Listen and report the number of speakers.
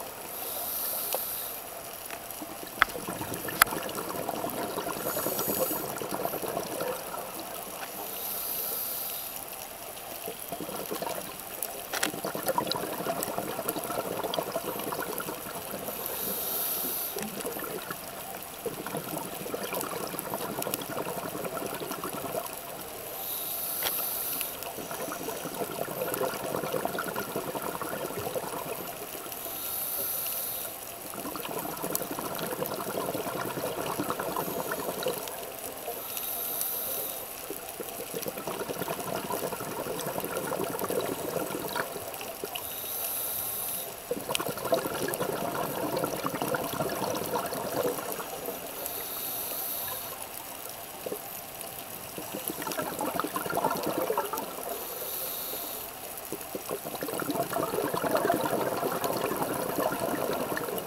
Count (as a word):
zero